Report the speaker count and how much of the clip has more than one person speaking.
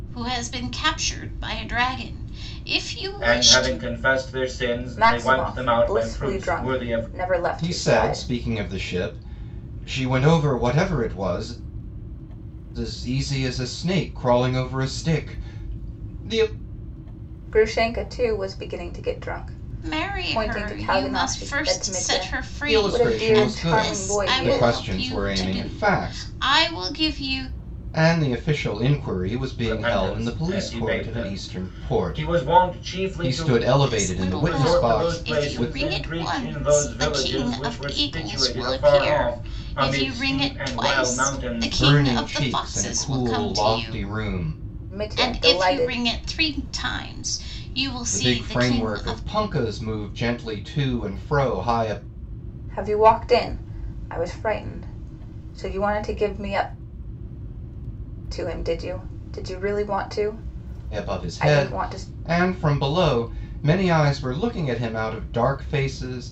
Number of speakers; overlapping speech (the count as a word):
four, about 41%